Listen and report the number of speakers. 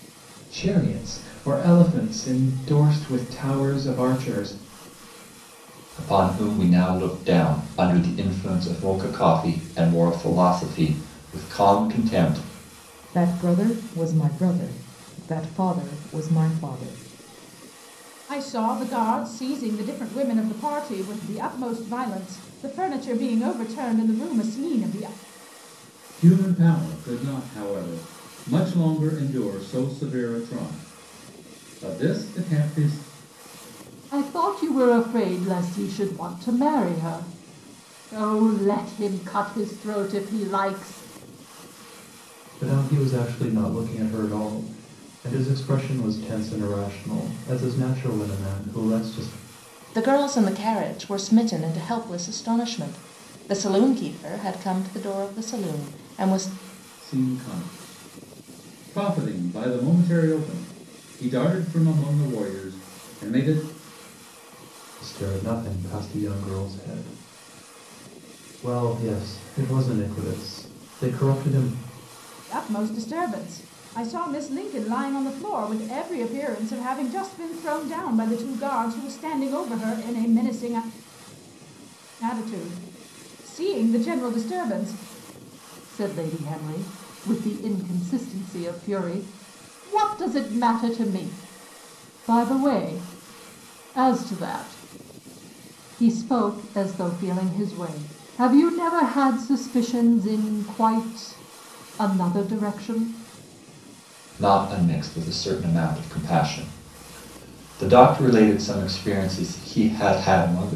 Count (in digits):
8